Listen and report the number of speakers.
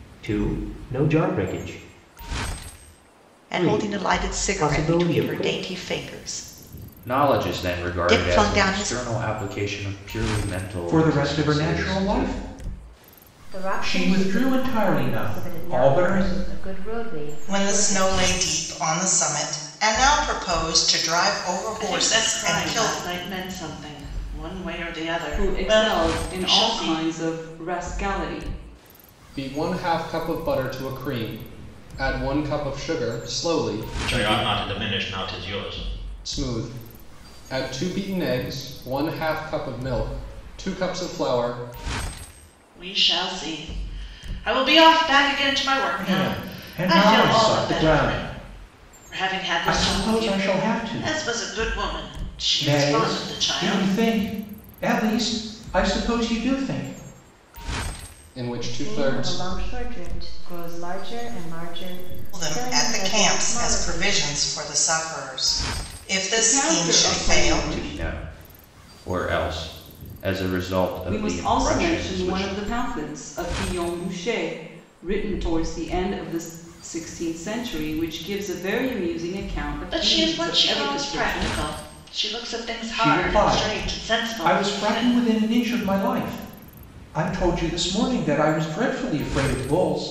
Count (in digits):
10